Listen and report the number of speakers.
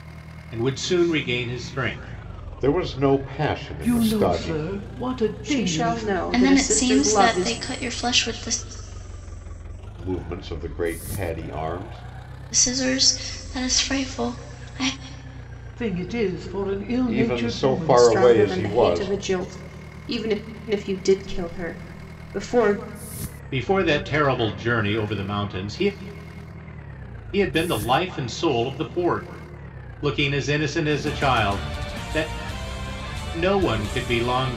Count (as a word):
five